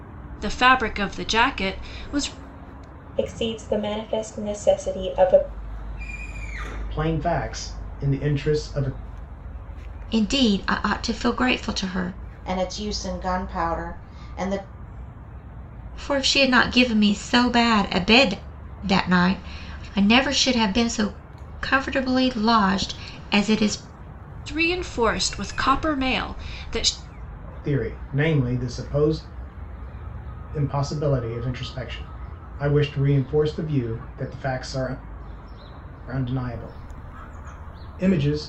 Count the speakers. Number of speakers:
five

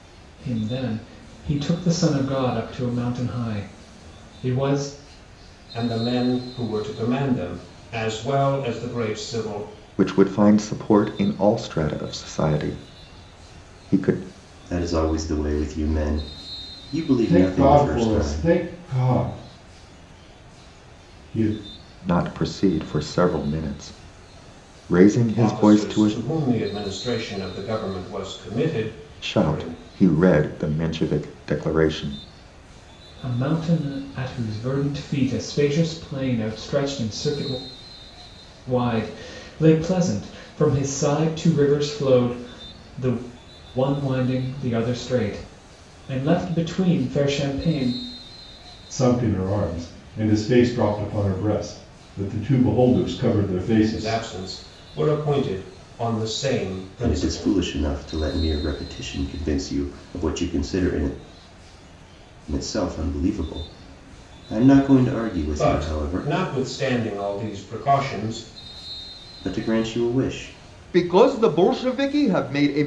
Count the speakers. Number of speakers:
five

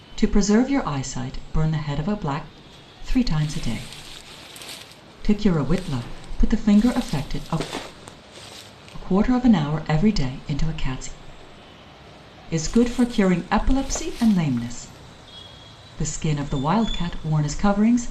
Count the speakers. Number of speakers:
one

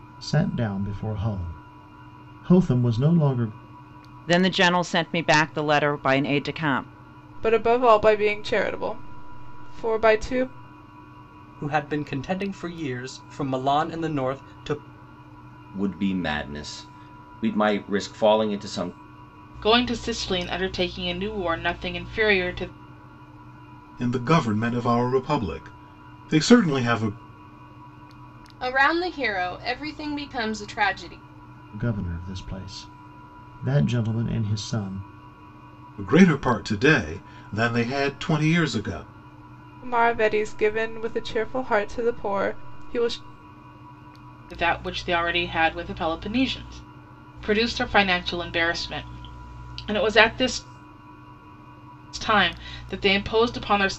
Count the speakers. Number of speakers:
eight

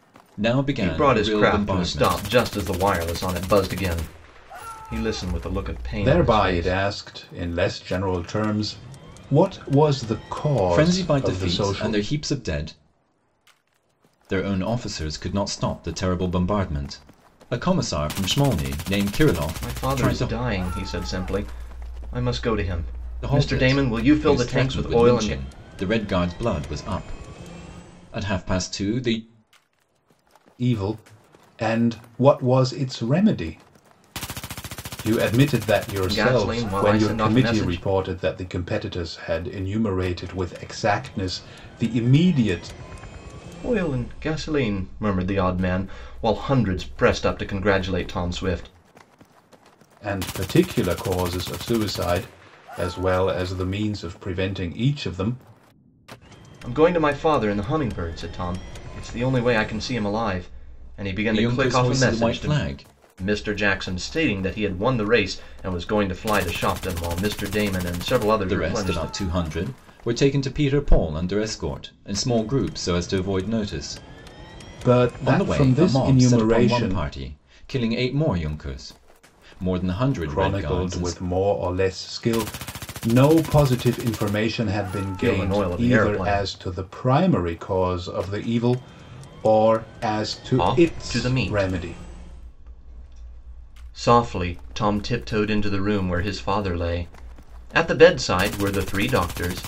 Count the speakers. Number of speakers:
three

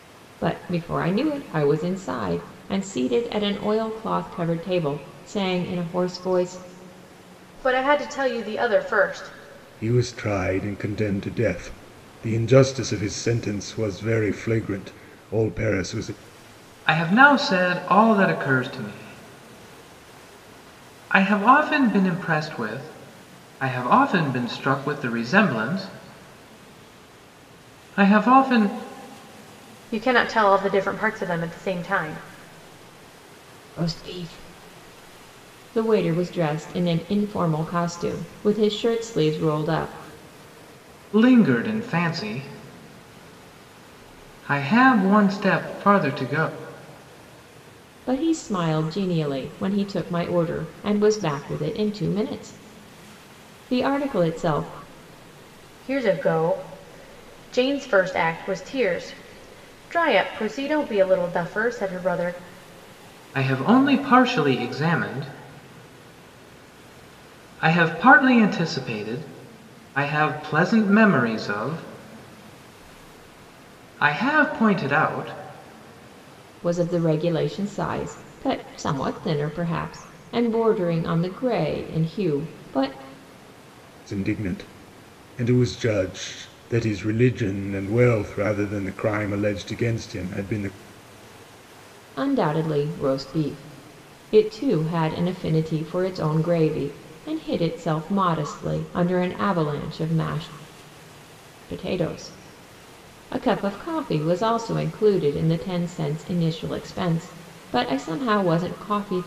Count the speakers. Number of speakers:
four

